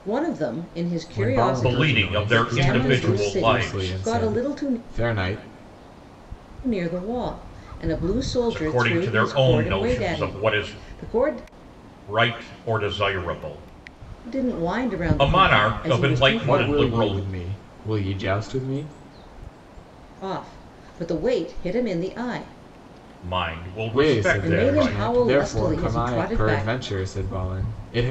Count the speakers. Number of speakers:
3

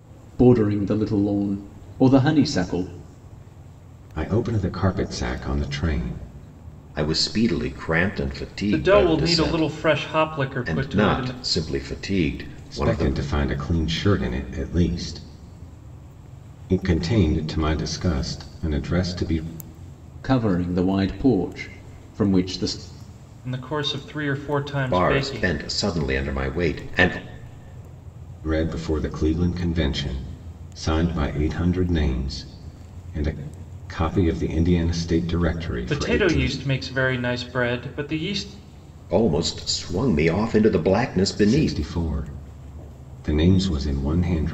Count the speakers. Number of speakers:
4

